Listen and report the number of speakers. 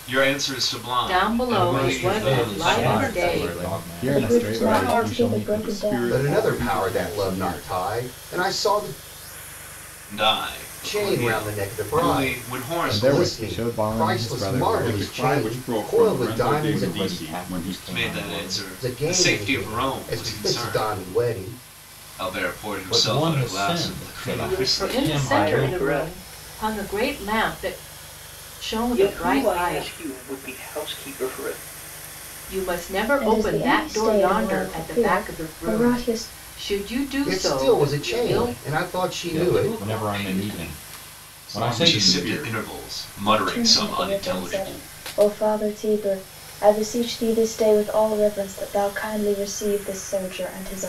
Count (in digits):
8